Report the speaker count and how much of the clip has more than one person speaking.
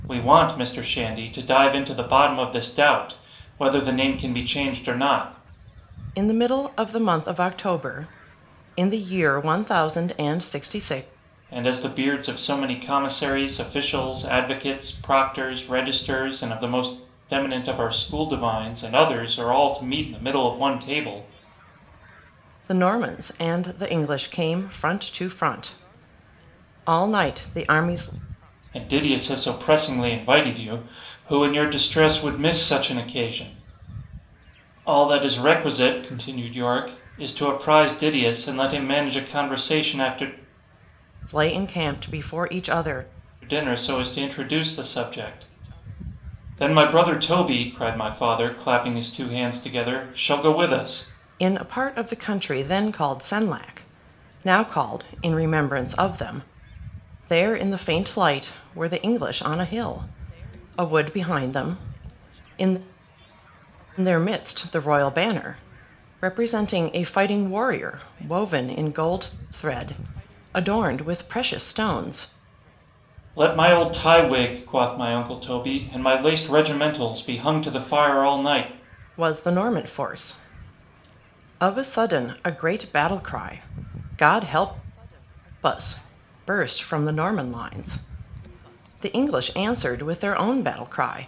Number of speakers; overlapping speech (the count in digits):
2, no overlap